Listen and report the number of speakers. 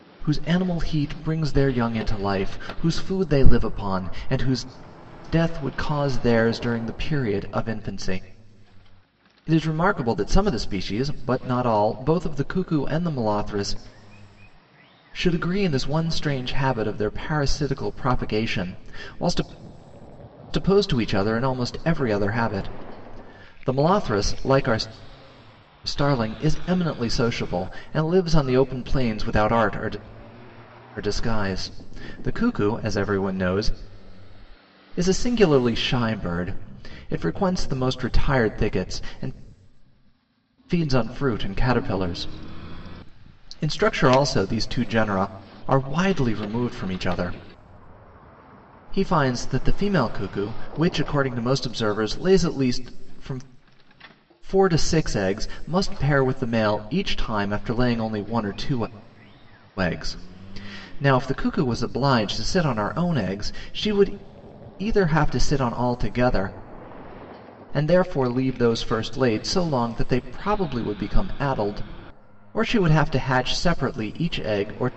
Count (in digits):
1